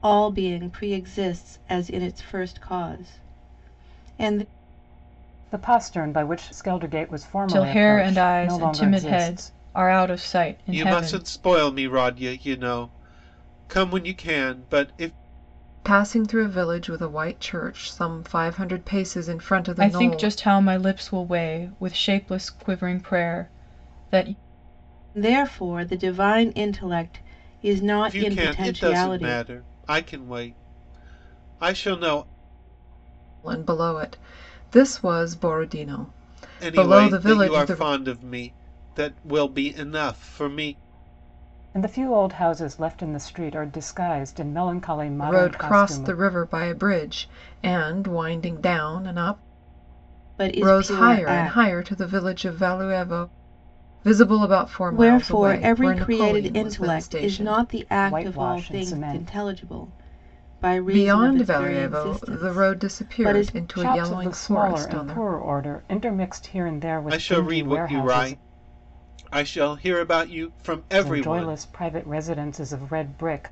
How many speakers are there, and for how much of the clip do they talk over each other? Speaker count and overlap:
5, about 25%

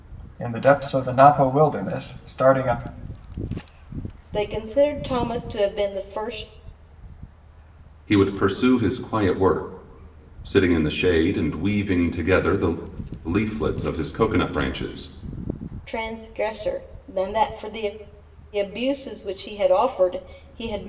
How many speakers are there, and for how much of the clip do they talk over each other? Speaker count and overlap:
3, no overlap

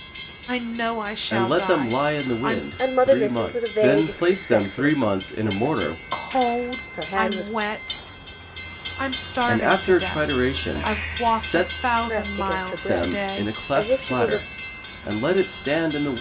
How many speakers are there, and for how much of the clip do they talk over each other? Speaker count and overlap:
3, about 65%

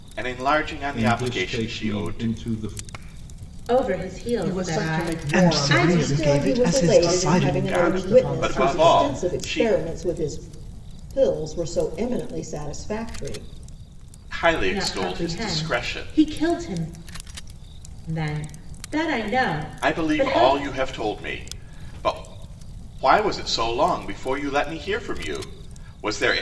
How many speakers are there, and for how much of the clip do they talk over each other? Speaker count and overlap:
6, about 34%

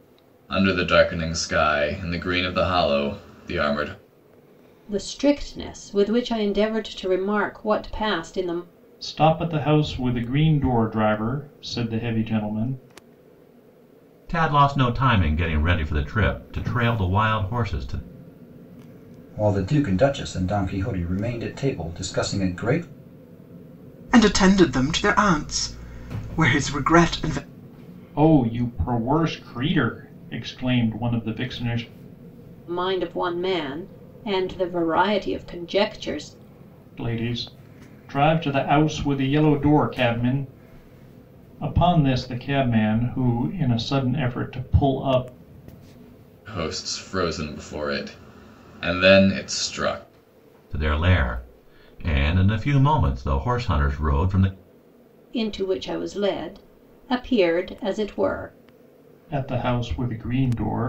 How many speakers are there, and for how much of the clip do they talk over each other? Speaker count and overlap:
6, no overlap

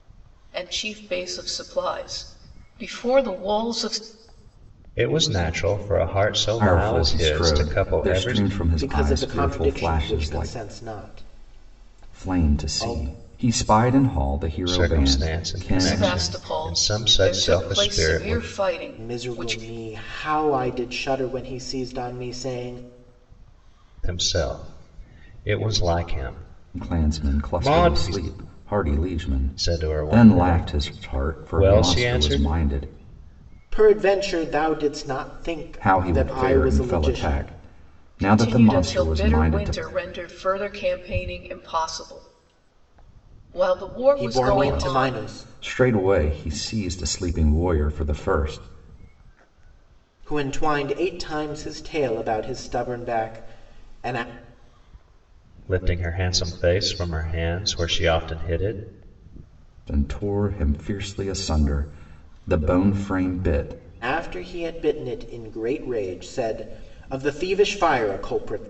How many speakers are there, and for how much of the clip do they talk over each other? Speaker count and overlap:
4, about 26%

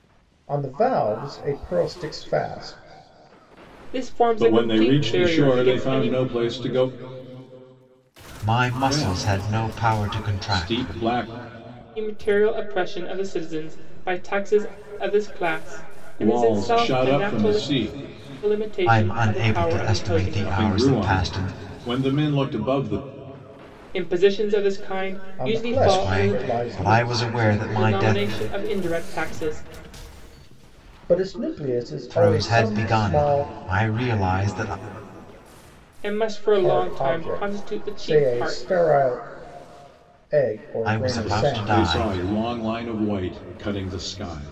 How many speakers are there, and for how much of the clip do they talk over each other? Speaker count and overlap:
4, about 34%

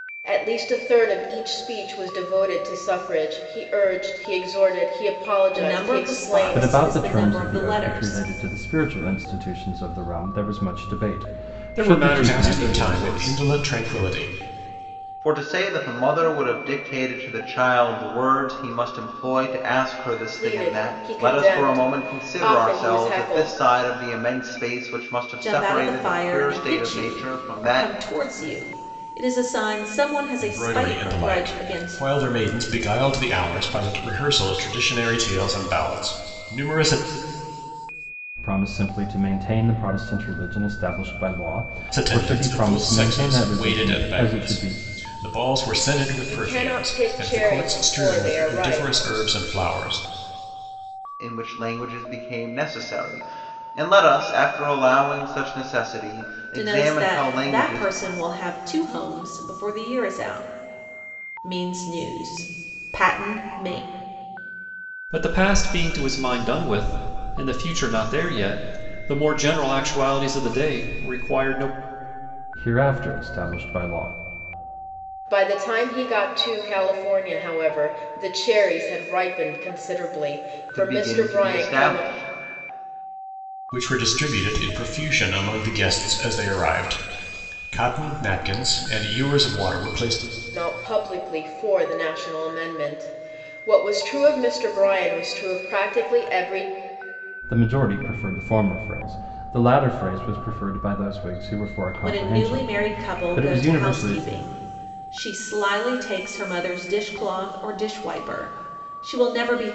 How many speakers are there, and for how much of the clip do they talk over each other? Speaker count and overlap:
6, about 21%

